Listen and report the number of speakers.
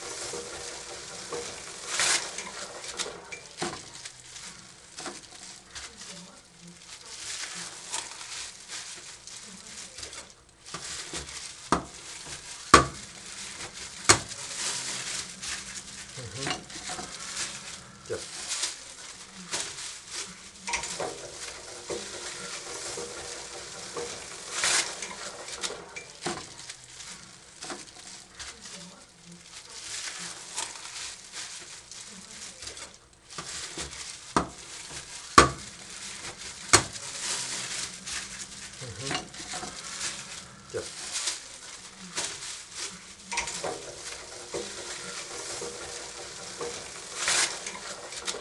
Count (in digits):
0